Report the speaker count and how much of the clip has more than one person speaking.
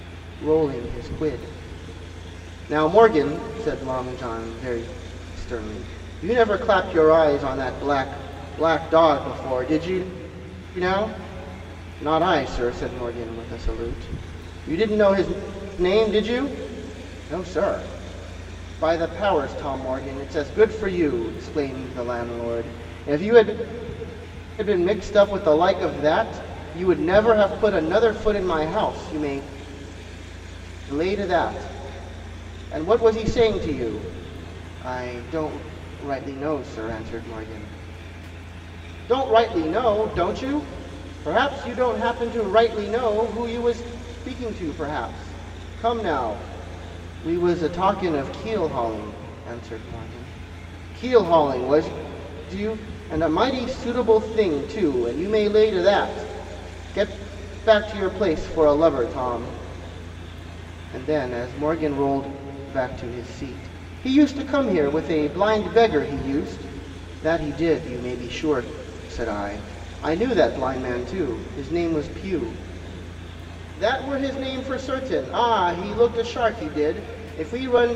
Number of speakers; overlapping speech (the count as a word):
one, no overlap